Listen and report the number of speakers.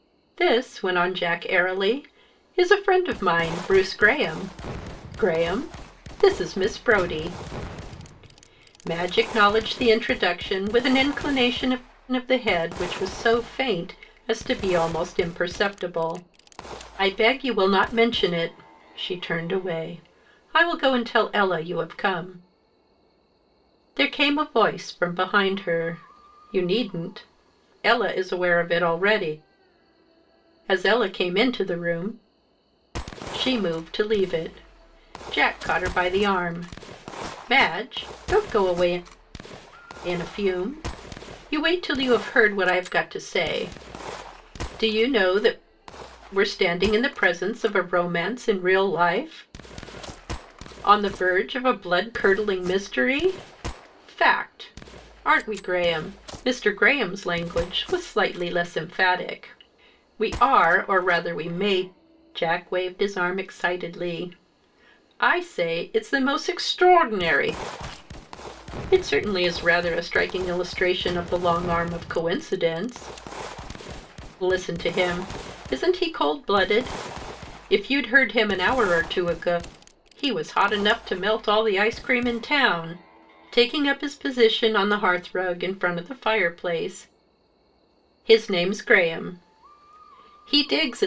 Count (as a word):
one